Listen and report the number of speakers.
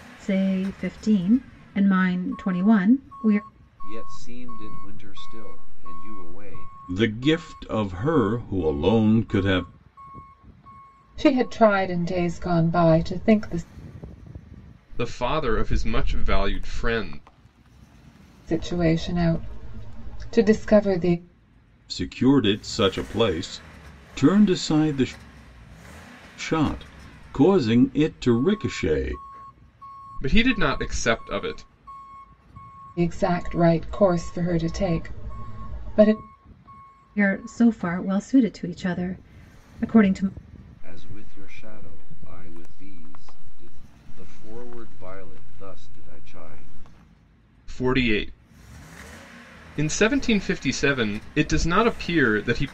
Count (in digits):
5